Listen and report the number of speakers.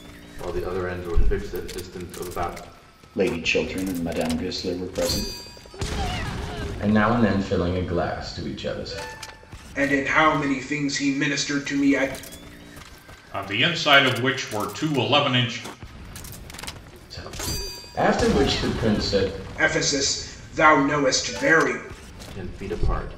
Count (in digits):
5